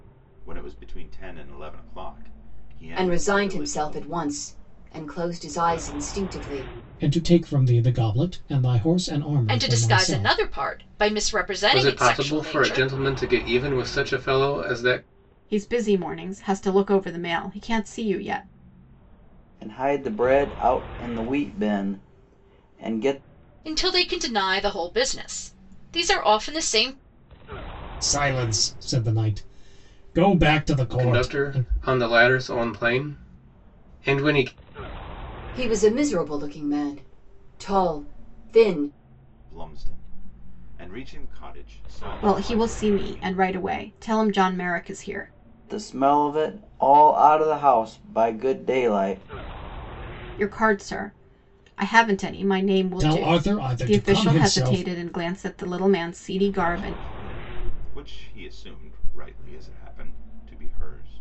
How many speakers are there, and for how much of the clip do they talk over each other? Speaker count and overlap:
7, about 12%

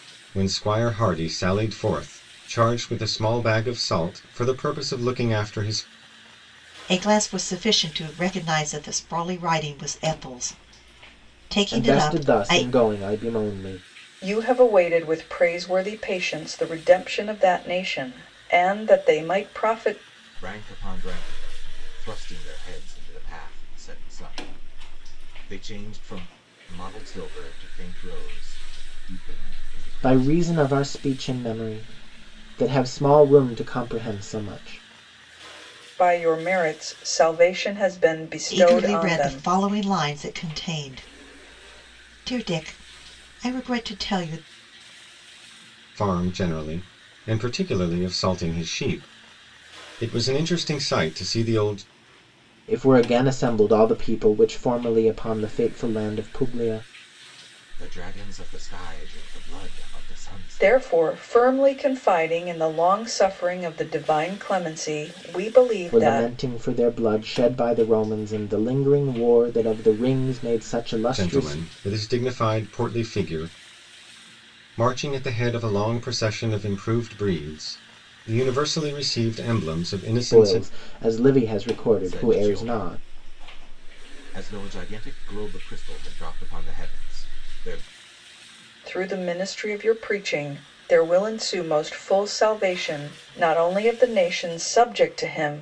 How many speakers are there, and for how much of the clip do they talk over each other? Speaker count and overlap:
5, about 6%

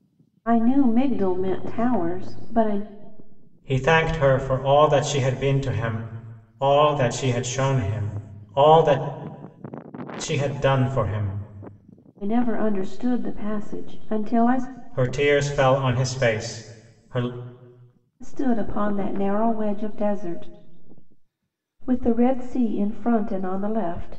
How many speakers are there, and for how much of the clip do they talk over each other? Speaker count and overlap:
2, no overlap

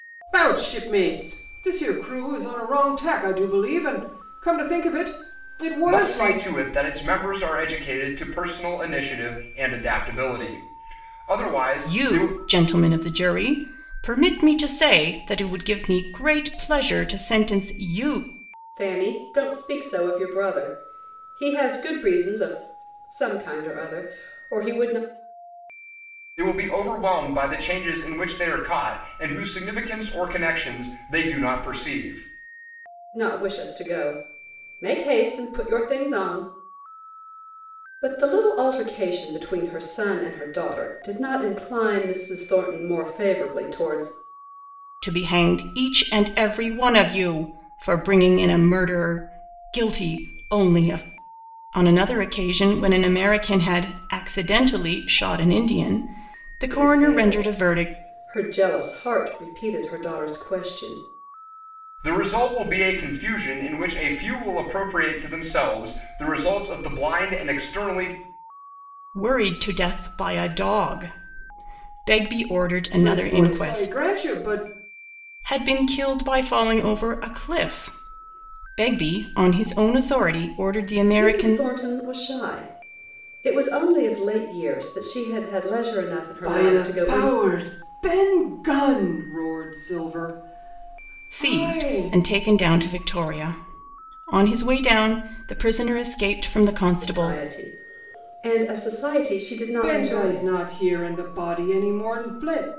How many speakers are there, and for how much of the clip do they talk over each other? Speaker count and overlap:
4, about 7%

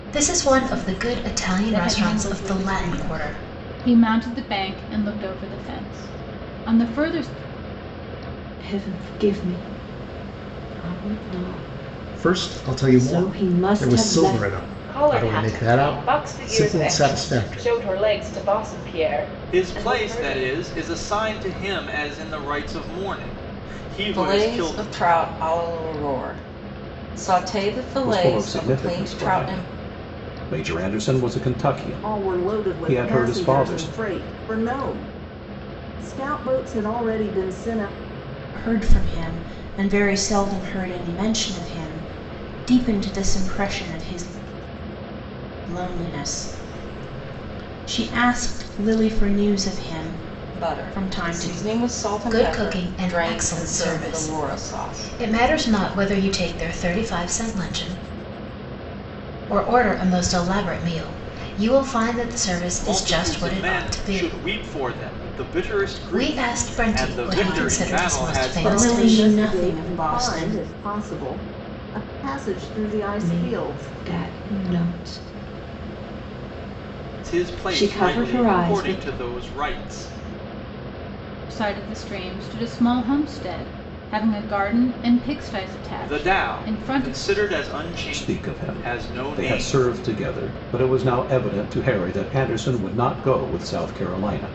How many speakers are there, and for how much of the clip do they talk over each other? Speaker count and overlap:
10, about 30%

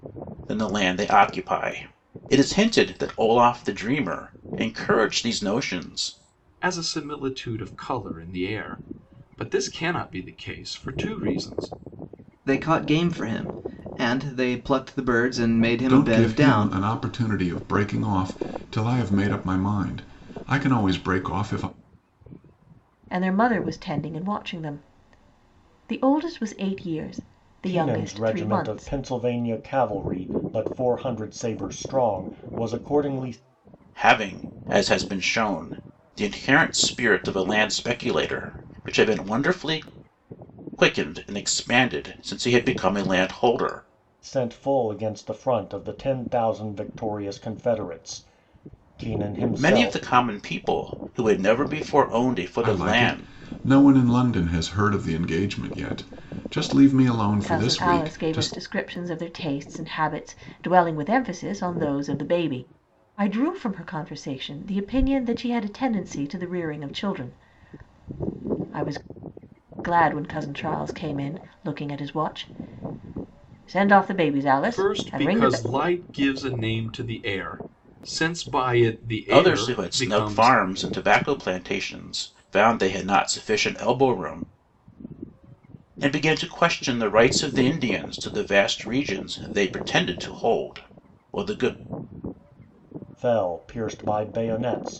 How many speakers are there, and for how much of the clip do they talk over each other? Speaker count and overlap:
6, about 7%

